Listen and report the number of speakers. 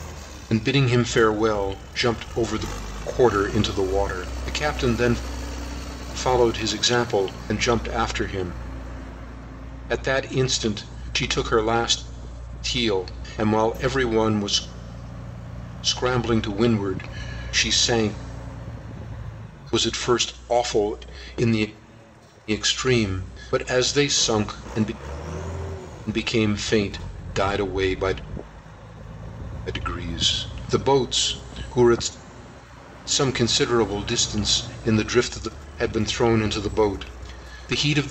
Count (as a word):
one